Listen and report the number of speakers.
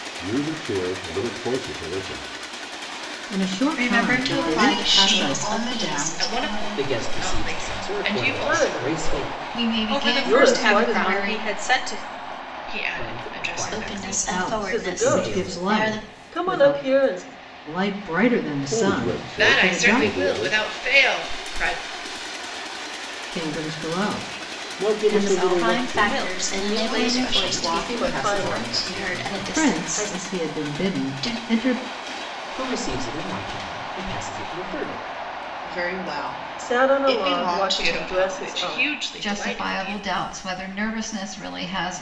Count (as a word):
ten